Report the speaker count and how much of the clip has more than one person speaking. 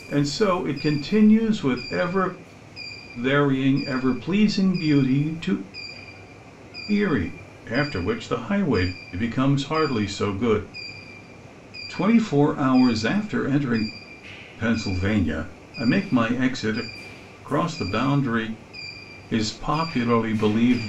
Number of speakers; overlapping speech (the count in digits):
1, no overlap